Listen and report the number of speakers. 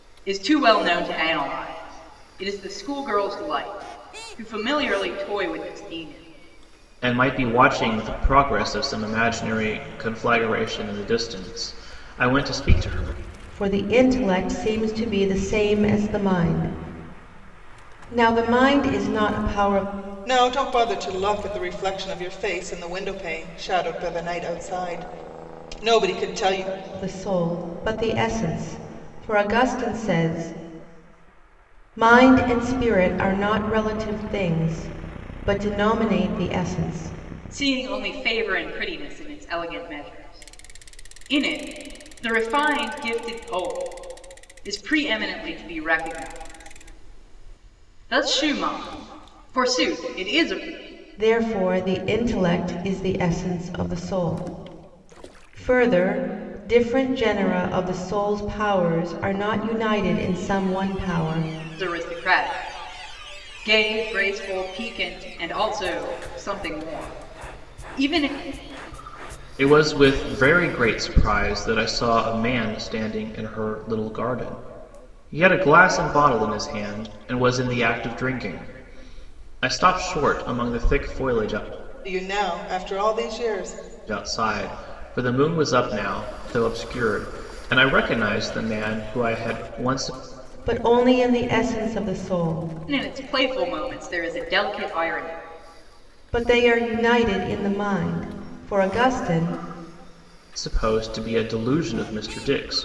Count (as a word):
four